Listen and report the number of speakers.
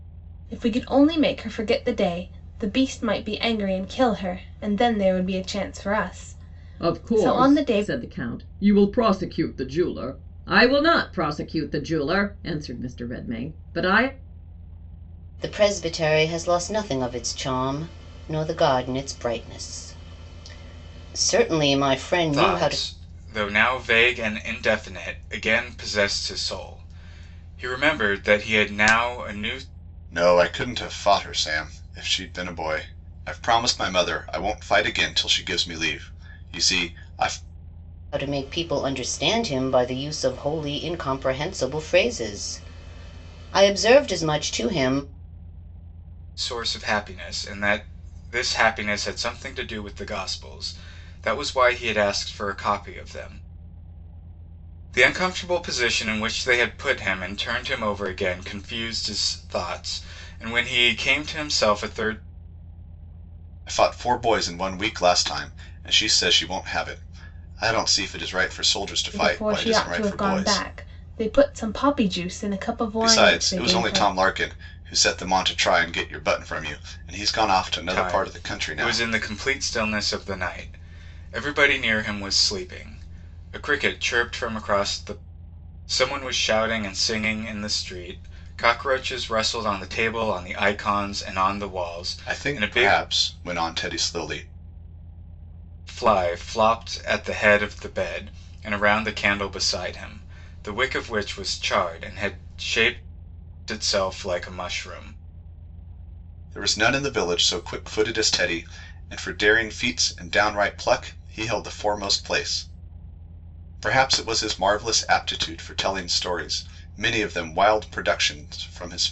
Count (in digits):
5